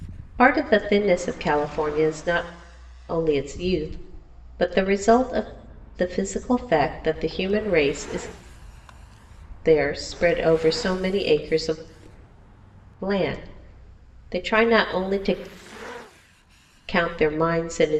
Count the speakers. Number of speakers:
one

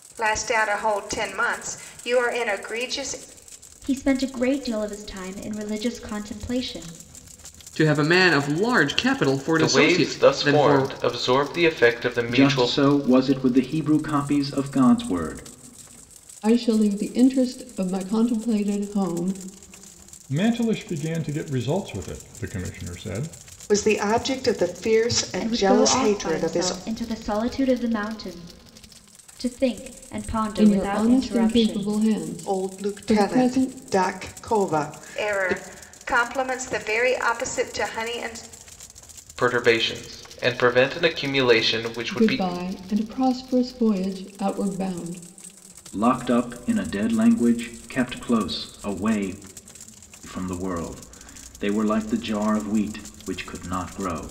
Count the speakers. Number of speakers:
eight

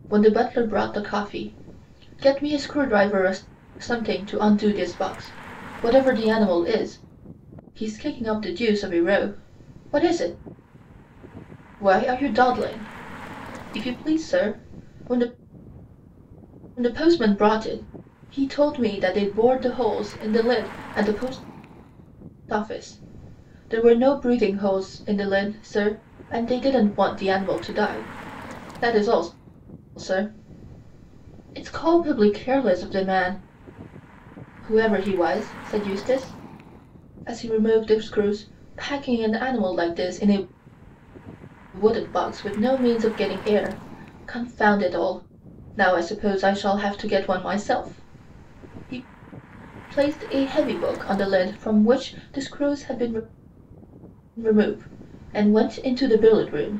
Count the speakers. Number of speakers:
one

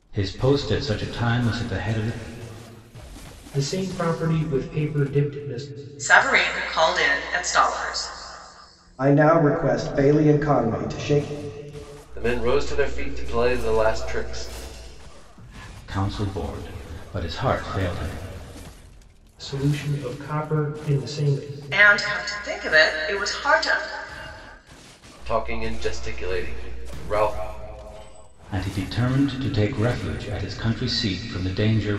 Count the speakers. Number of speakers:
five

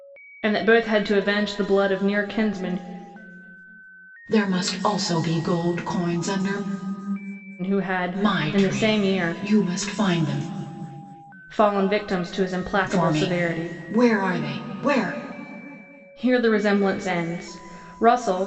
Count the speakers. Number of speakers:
two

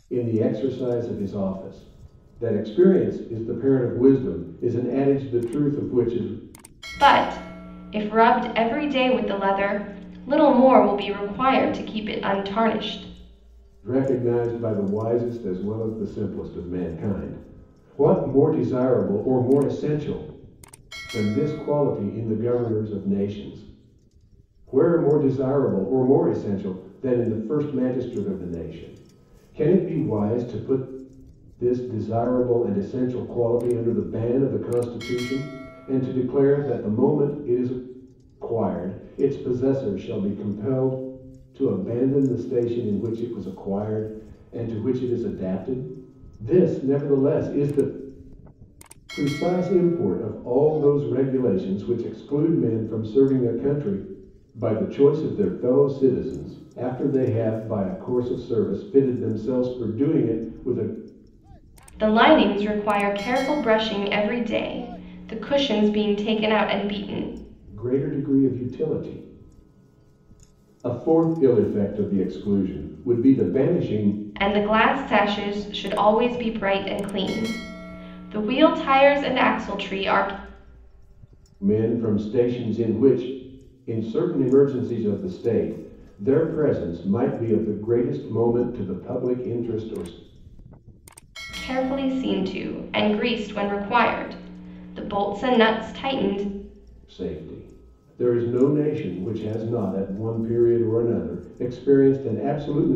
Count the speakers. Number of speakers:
two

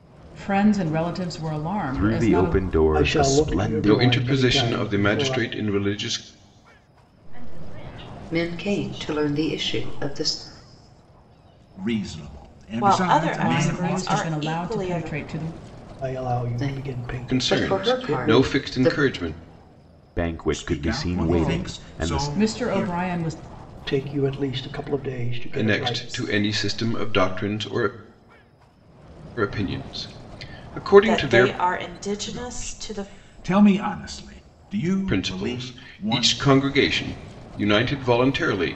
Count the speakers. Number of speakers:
eight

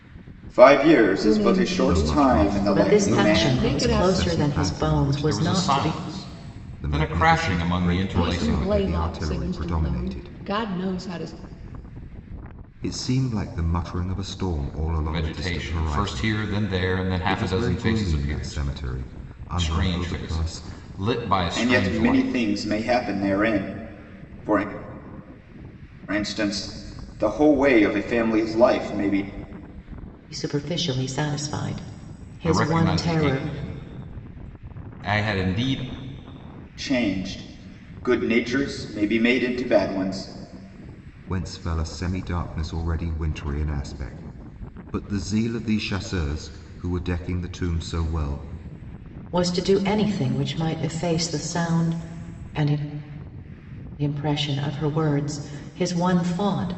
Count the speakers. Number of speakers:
five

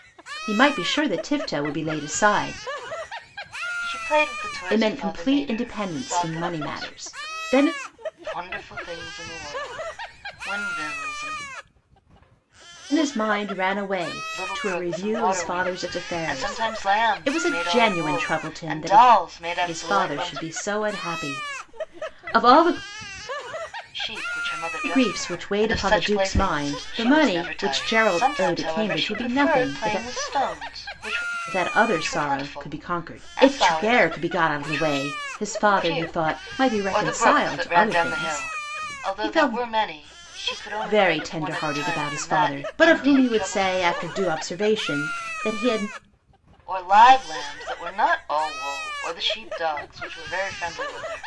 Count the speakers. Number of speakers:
two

